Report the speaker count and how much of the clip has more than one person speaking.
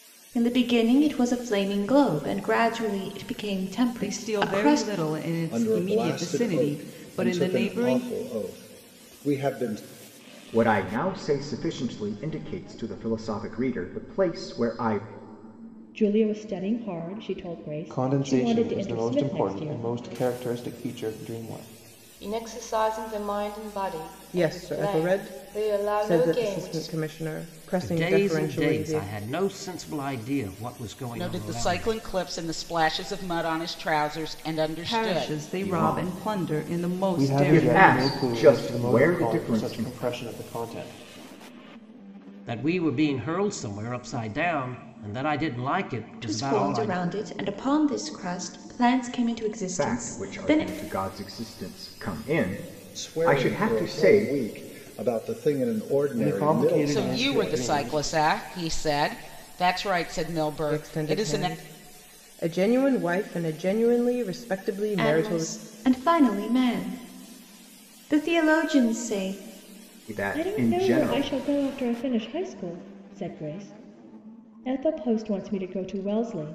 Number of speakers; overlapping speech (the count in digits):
10, about 30%